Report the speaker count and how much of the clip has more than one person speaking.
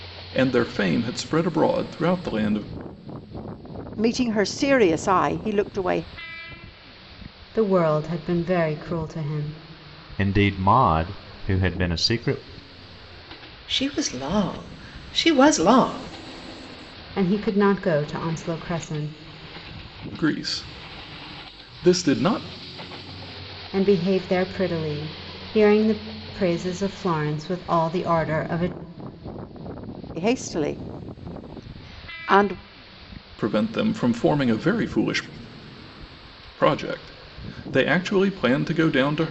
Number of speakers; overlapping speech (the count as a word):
five, no overlap